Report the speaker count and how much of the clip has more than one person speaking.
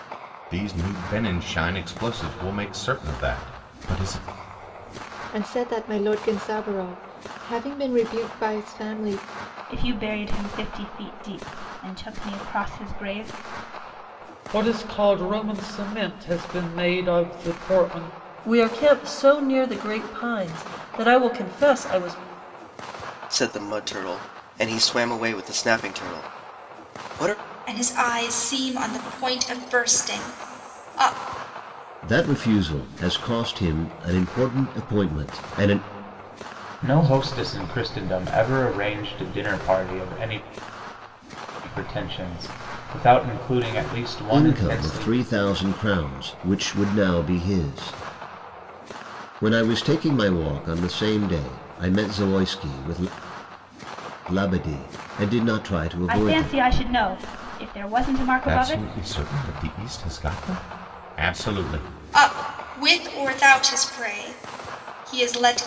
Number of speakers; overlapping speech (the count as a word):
nine, about 3%